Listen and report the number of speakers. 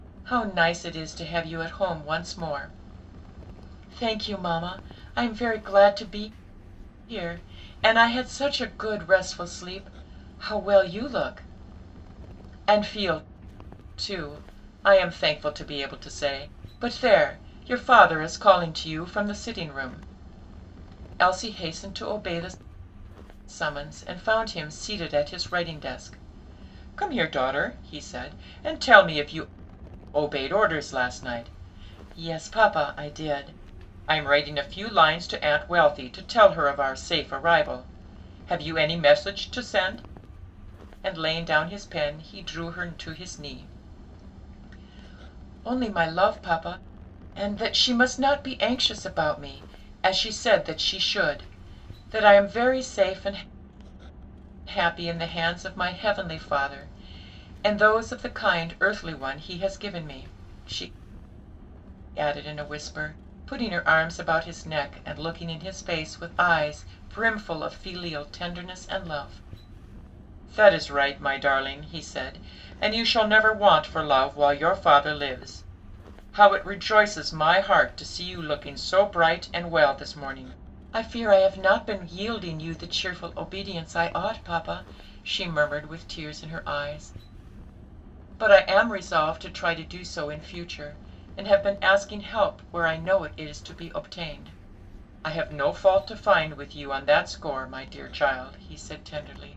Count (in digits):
1